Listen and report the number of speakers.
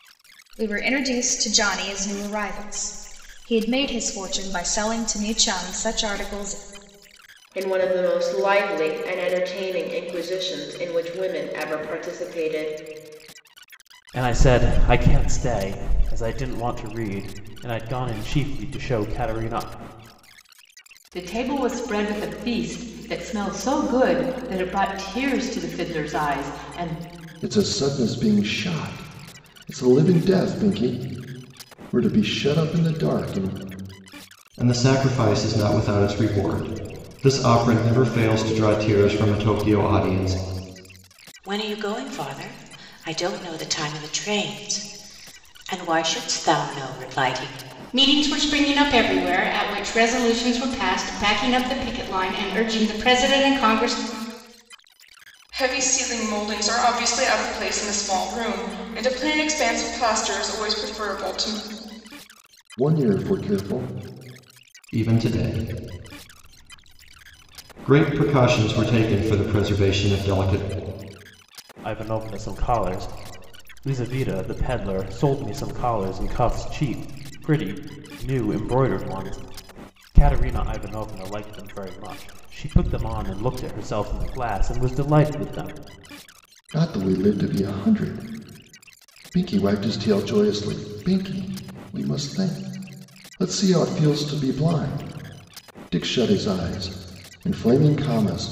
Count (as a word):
nine